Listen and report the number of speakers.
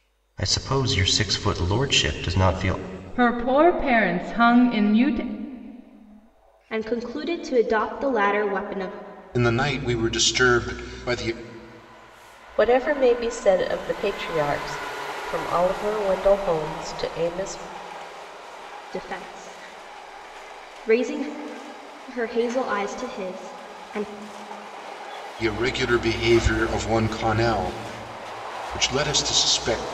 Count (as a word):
five